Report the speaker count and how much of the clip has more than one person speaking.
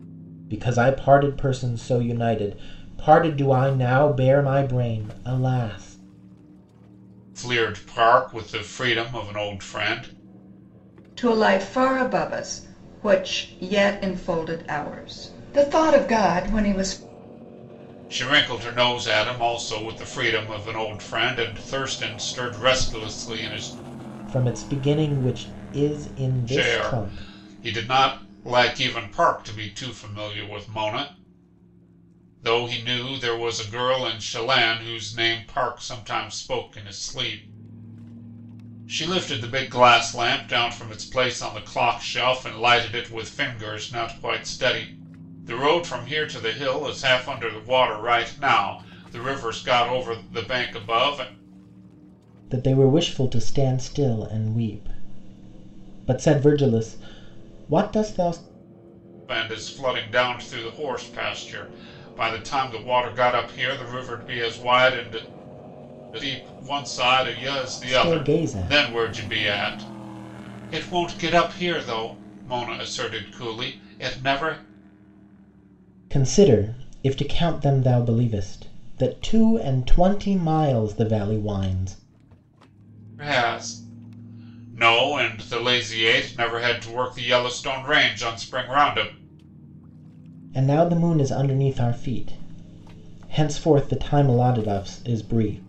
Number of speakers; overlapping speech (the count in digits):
3, about 2%